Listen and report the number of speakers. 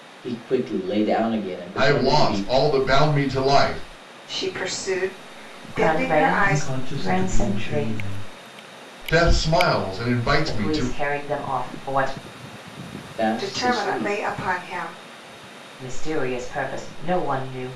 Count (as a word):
five